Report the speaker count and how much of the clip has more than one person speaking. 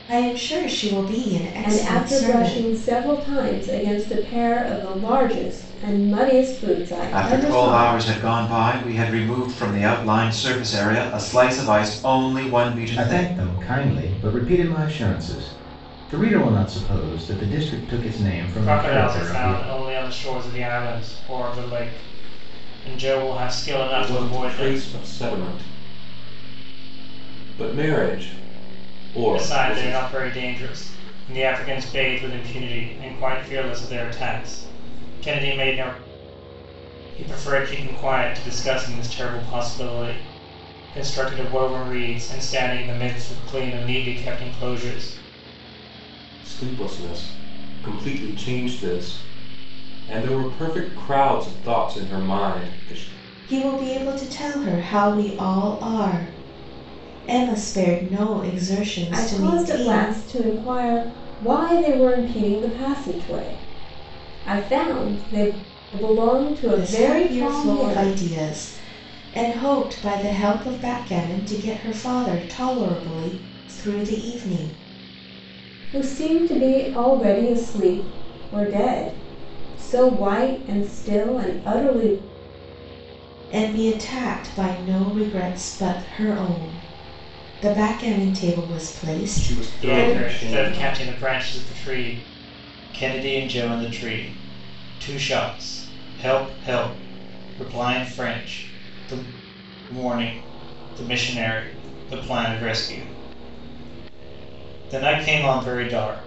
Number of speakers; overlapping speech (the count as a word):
six, about 9%